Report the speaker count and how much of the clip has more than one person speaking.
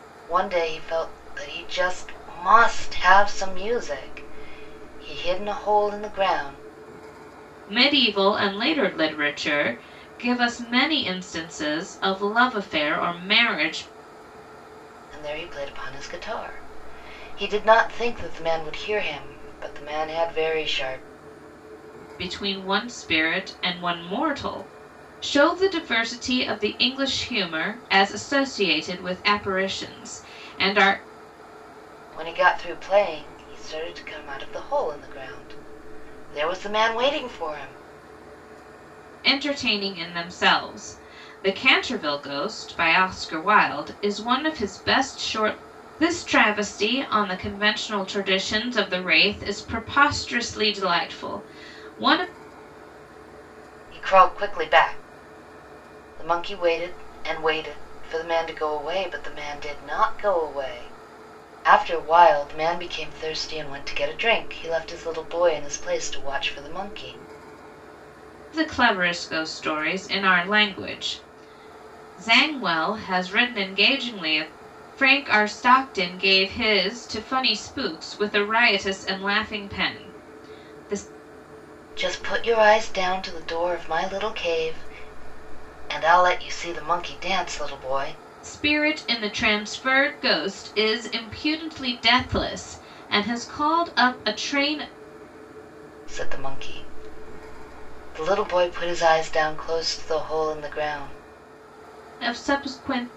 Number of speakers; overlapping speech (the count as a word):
two, no overlap